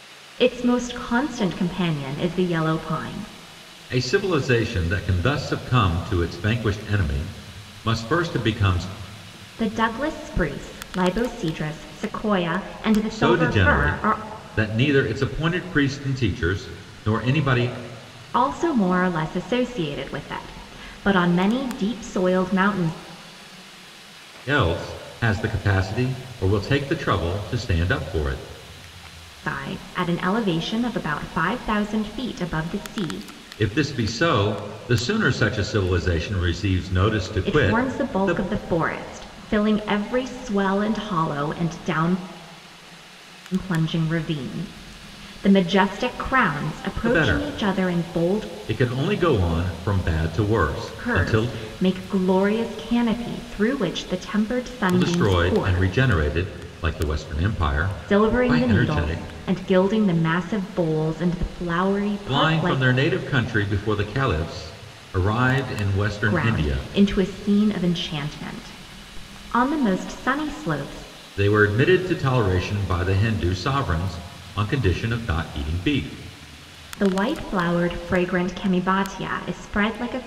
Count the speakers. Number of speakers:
two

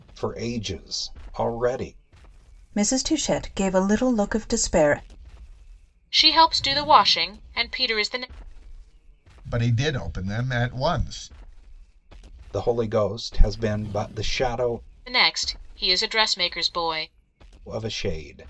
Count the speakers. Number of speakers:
four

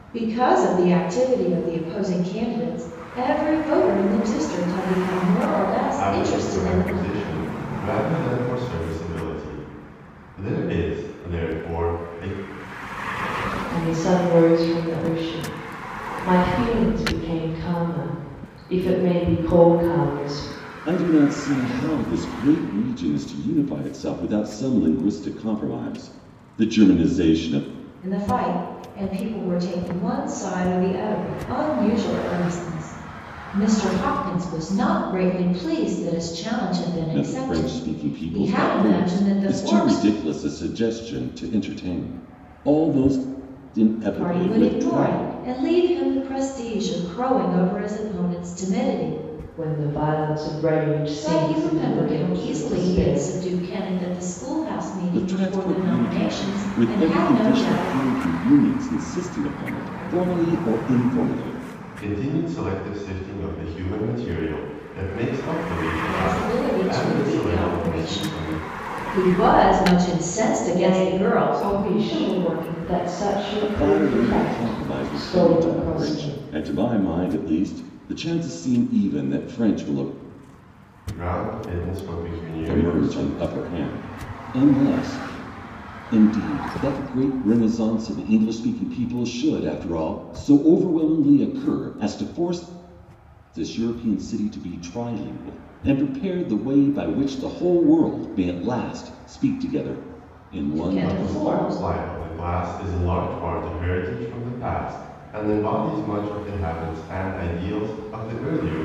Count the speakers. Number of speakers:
four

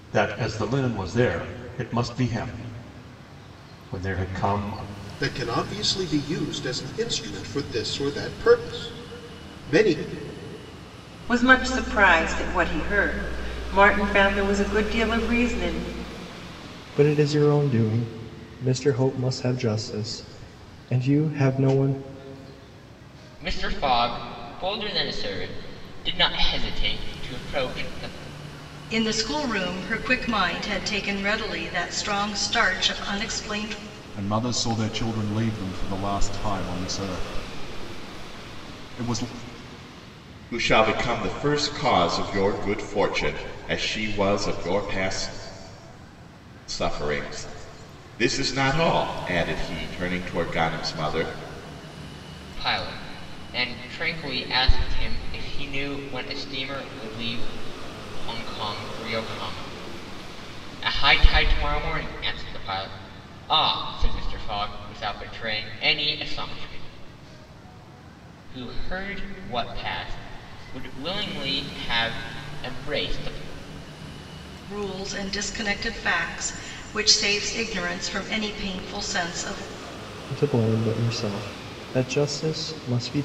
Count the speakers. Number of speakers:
eight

